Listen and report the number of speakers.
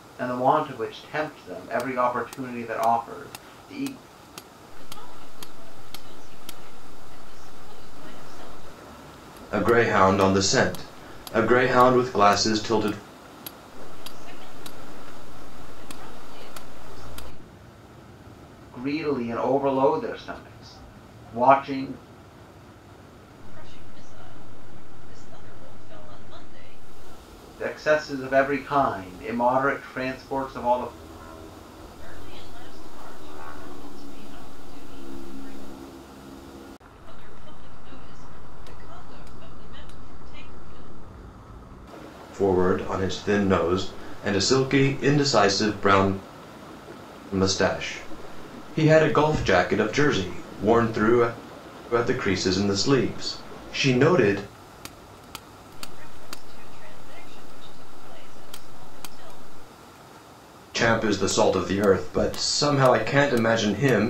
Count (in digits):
3